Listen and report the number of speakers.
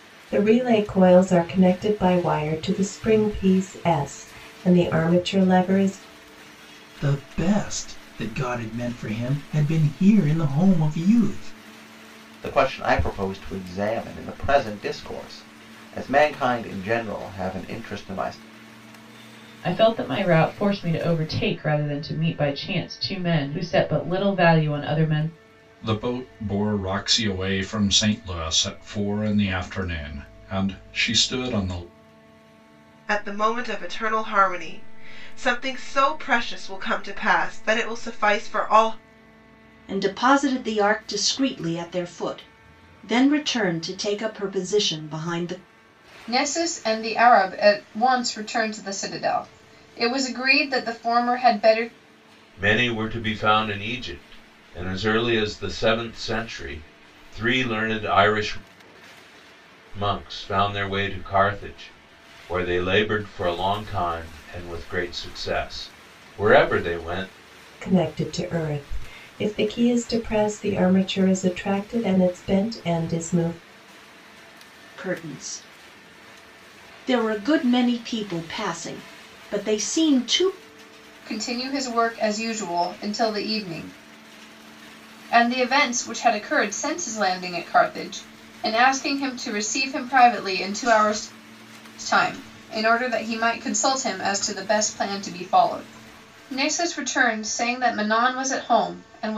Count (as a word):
nine